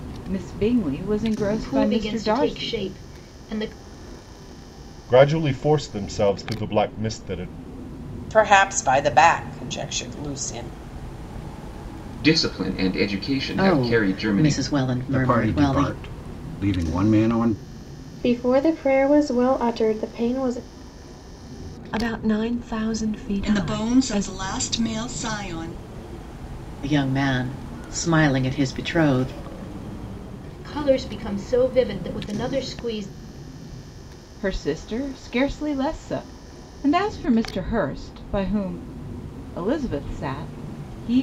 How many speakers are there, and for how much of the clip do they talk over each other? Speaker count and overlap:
10, about 10%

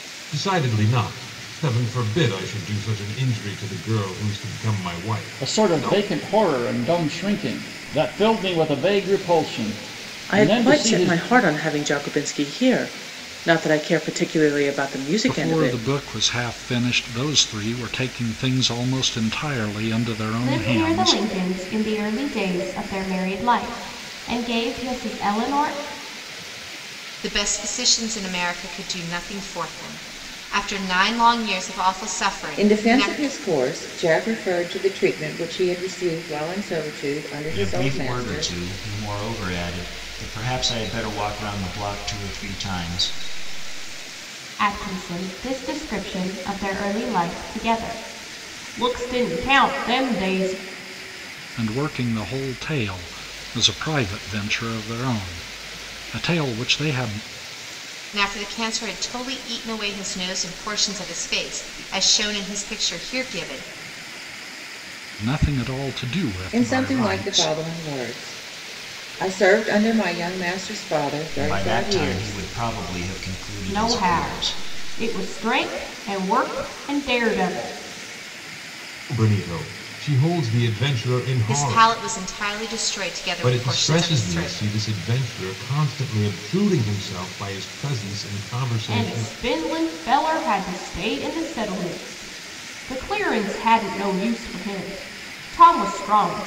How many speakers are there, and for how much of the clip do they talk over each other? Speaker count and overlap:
8, about 10%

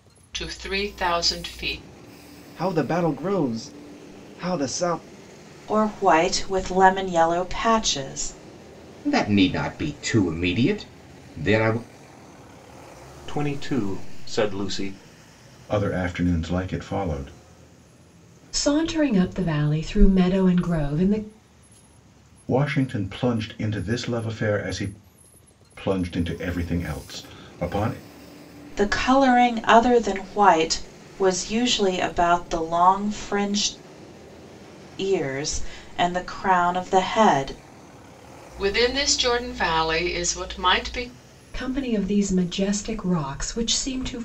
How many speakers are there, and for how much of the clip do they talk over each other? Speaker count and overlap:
7, no overlap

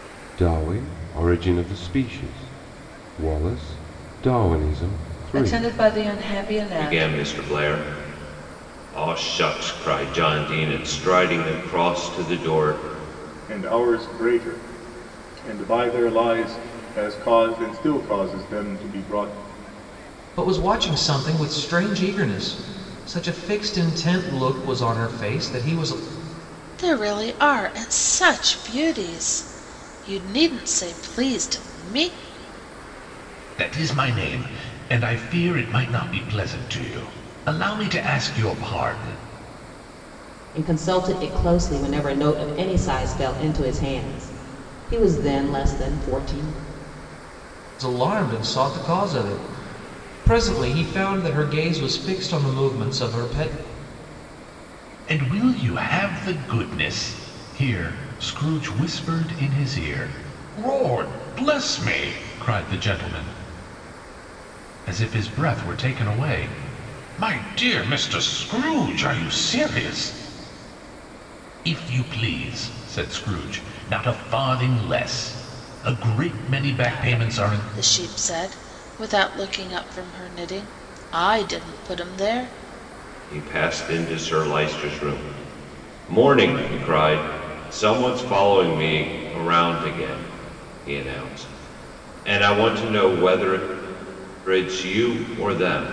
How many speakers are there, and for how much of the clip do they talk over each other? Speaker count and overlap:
8, about 2%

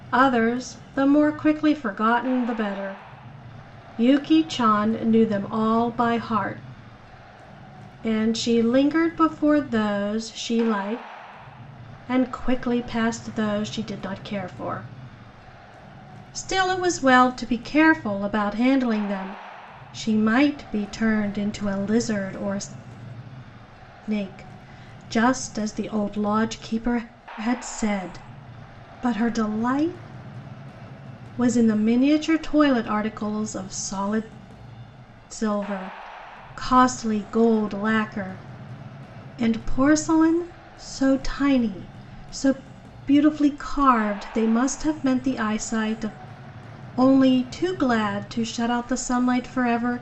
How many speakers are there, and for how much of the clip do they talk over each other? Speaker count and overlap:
1, no overlap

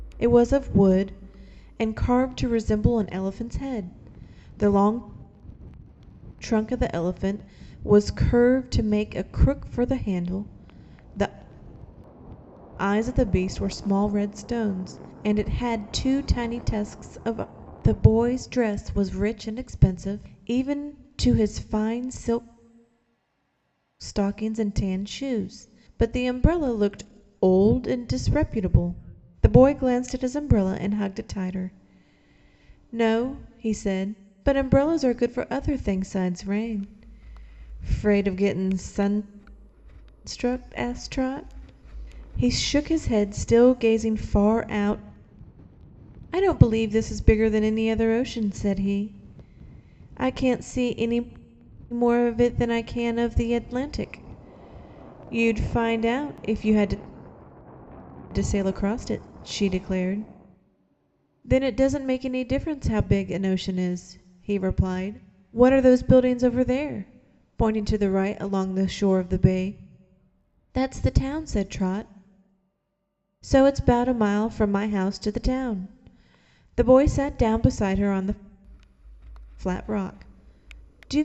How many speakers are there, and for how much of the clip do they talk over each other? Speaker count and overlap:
1, no overlap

